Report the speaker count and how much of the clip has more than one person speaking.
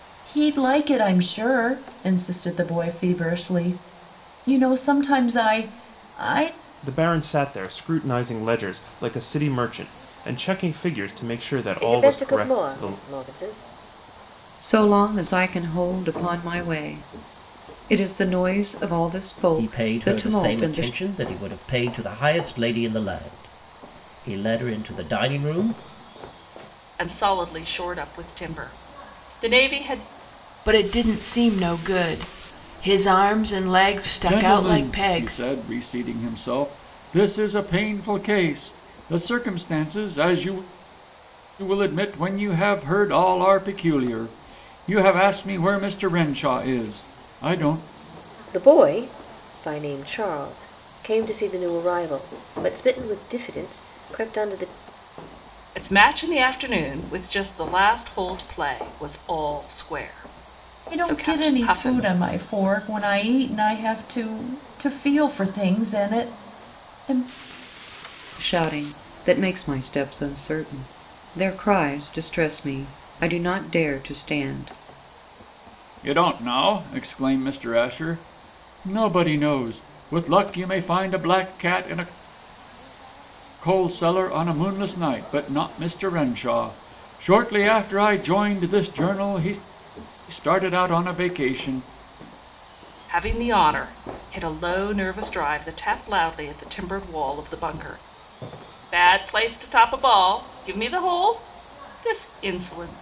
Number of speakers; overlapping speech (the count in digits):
8, about 5%